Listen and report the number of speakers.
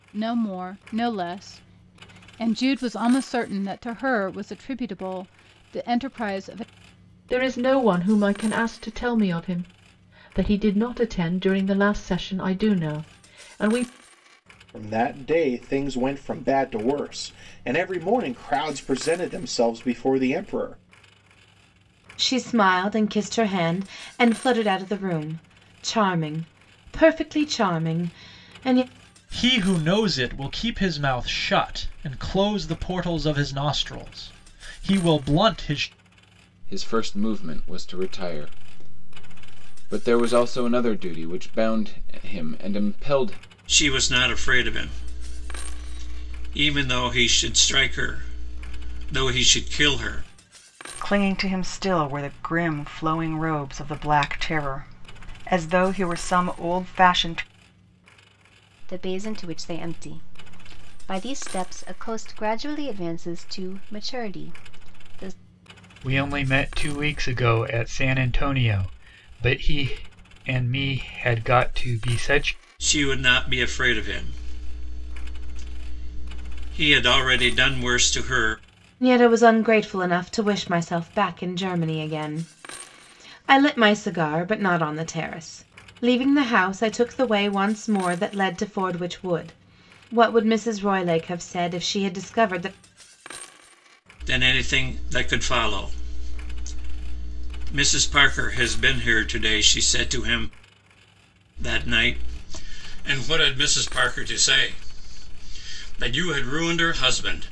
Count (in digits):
10